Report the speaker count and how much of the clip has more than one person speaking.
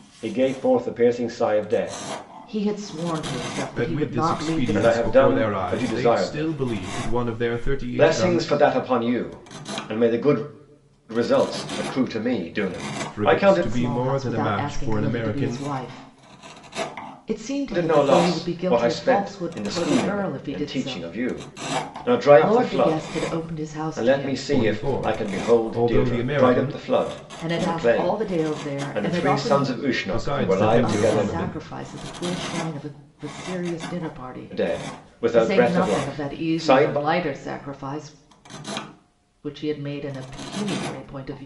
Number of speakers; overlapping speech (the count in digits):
3, about 44%